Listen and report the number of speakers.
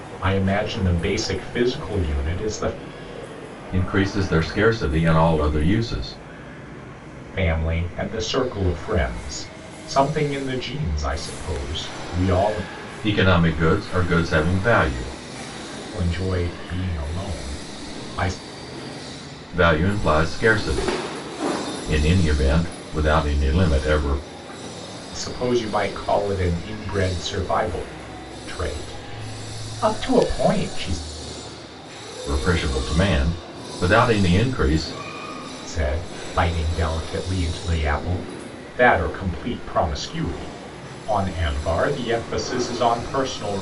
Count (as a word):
two